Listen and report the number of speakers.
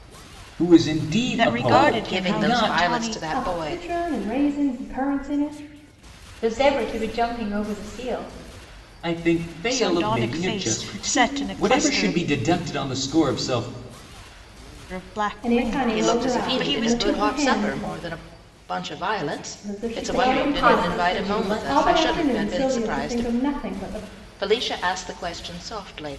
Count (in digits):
5